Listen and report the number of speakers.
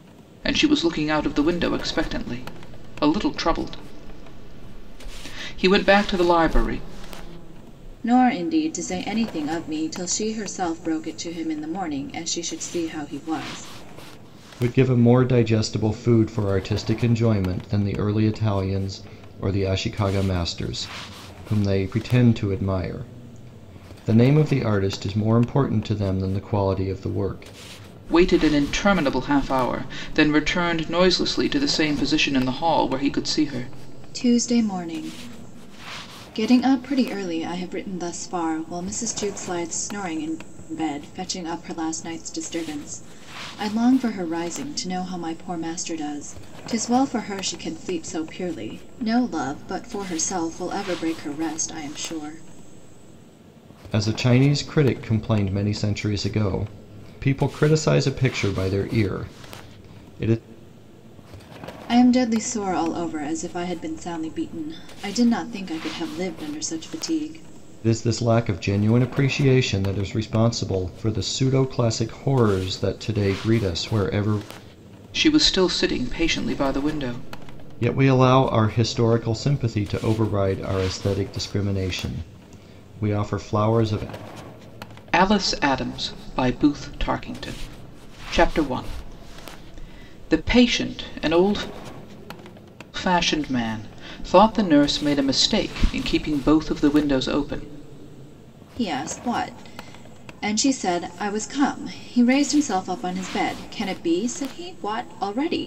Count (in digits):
3